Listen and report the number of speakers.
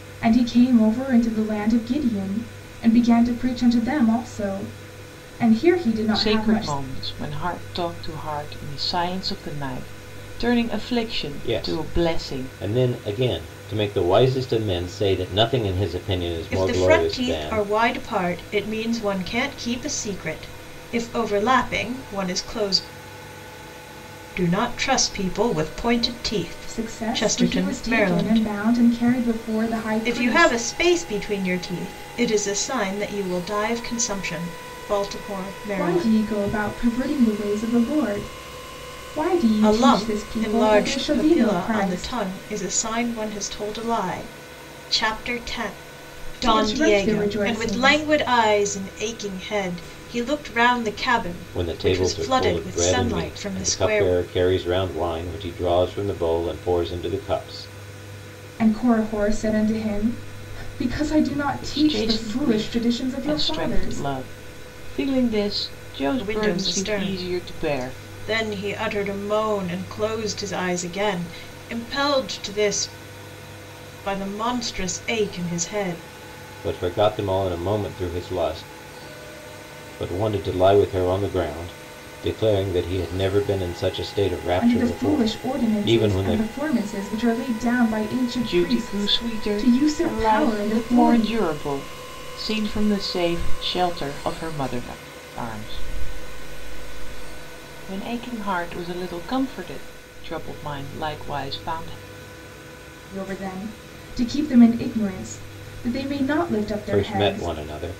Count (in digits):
4